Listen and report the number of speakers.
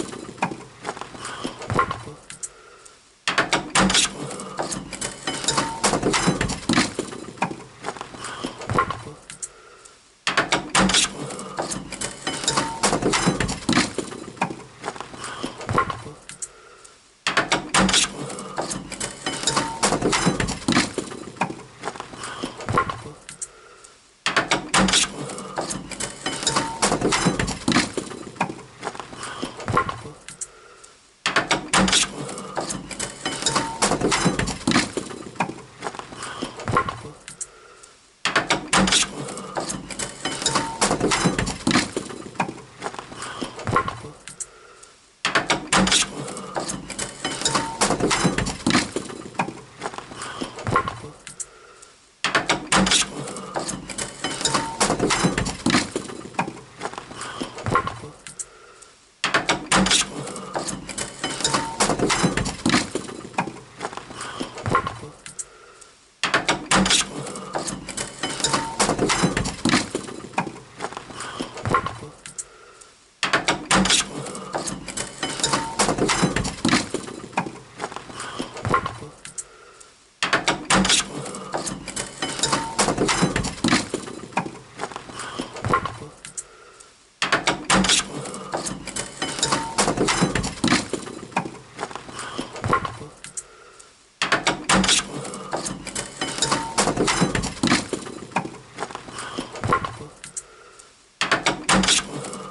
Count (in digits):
0